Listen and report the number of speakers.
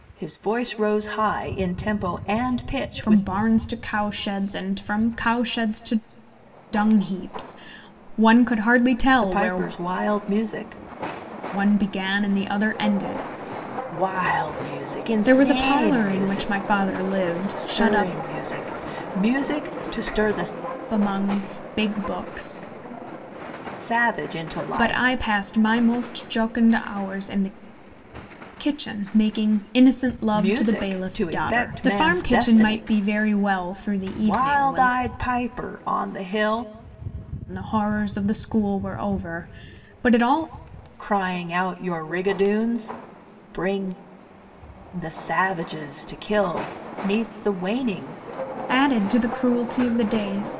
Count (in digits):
2